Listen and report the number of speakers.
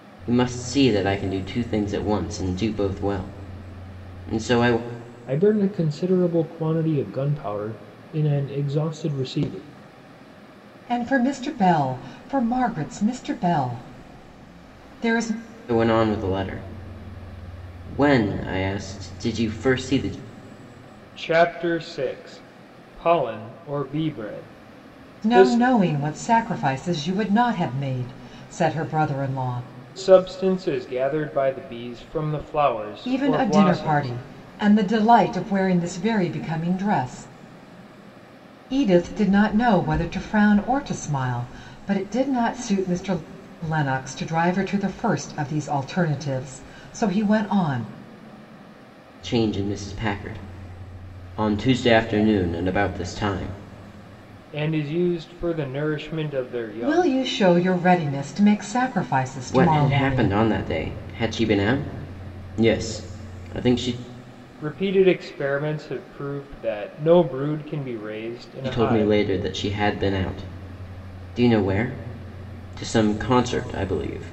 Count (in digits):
3